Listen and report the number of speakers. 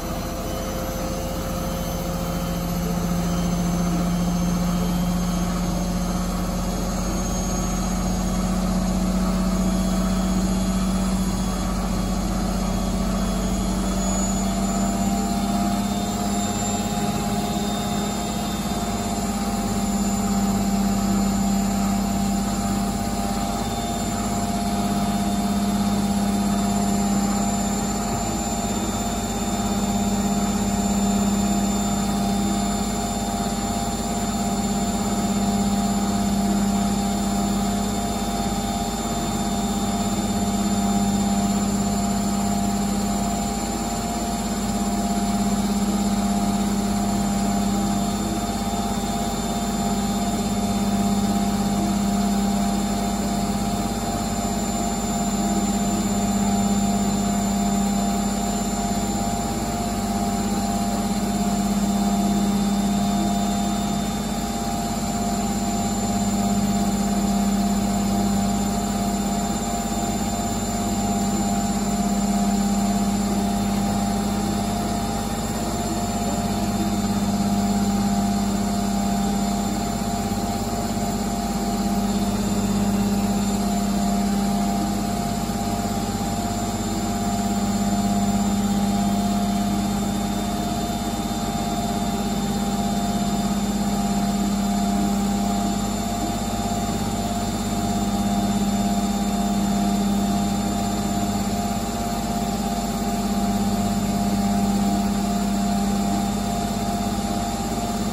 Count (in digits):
0